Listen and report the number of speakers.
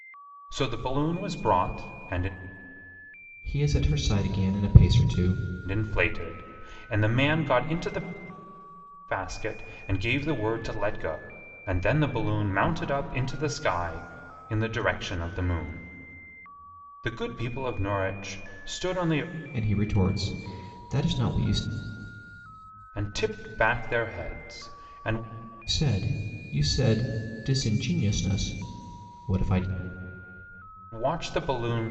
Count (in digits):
2